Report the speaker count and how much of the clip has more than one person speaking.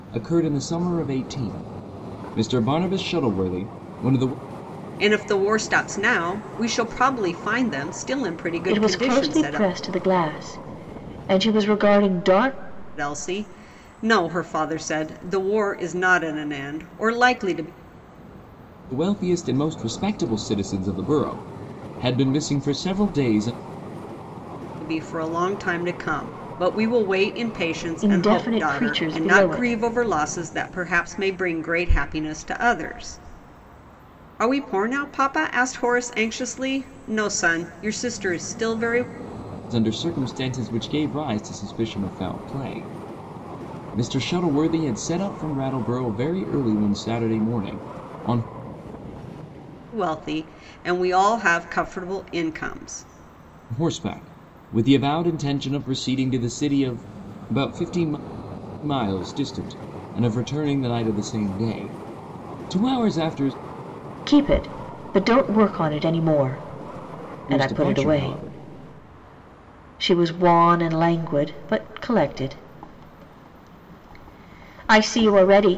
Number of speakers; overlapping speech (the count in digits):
3, about 5%